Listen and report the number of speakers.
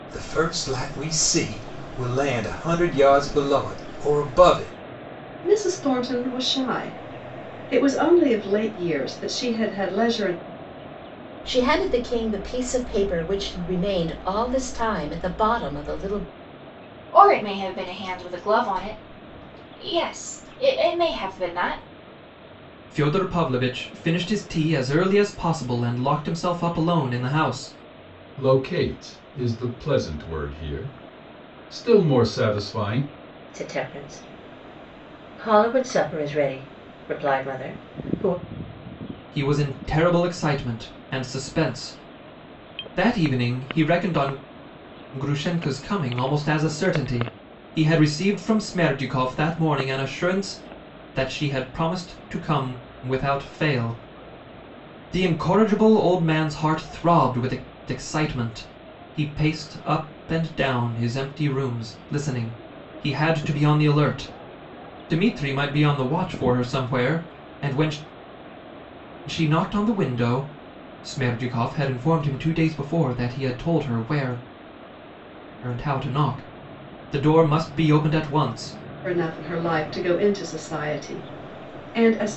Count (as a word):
seven